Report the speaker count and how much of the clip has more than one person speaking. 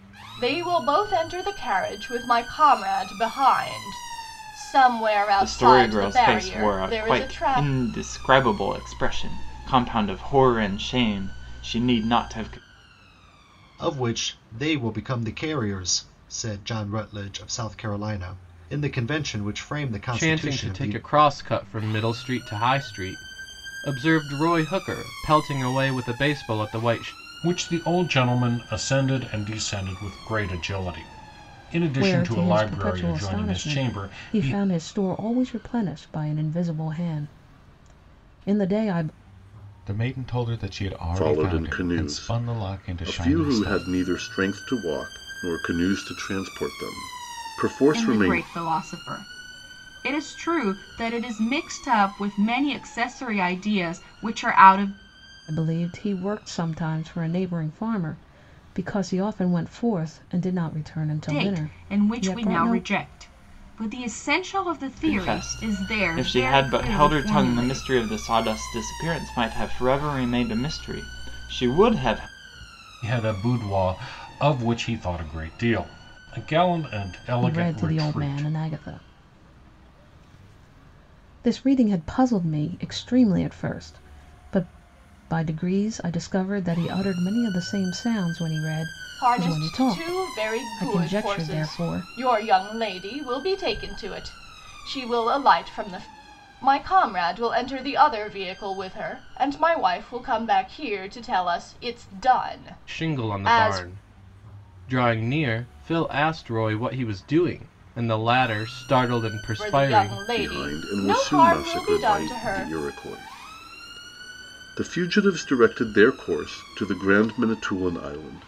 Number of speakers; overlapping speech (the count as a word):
nine, about 19%